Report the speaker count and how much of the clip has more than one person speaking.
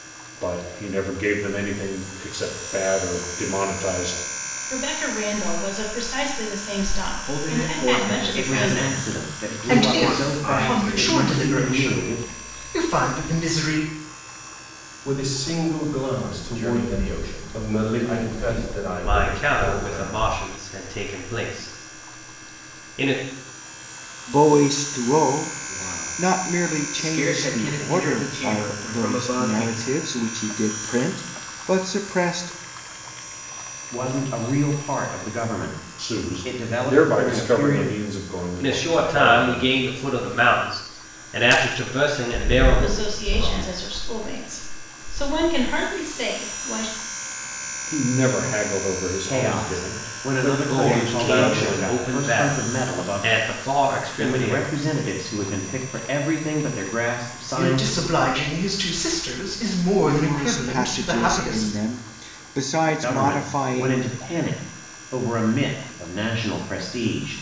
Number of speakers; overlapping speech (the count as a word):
nine, about 39%